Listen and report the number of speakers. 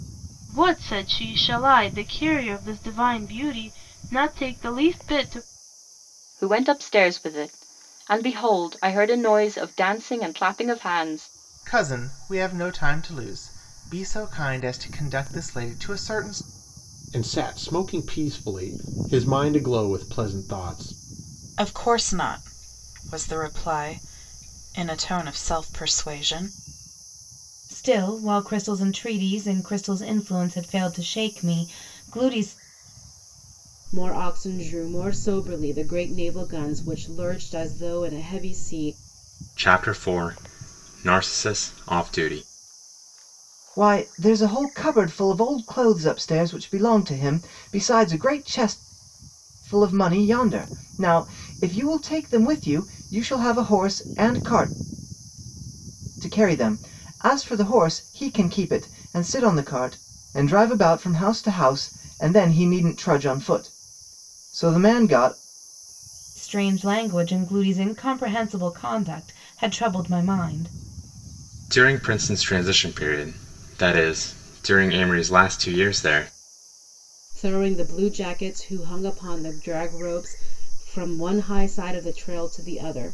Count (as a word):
nine